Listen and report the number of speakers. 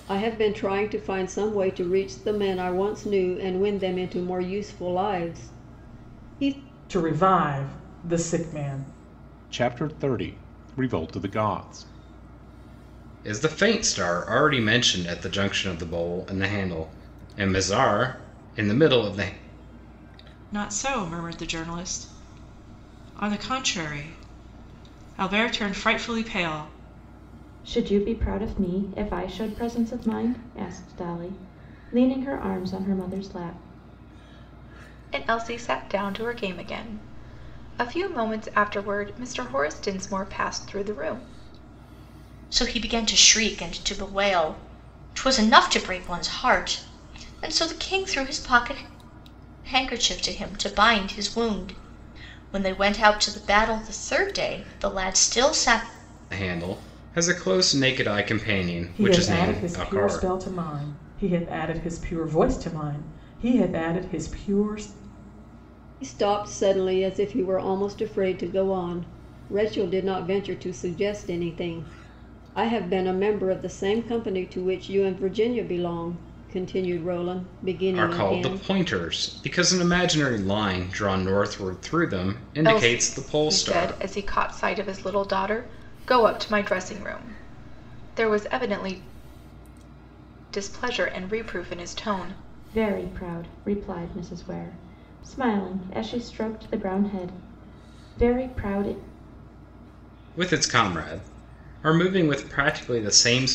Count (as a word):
eight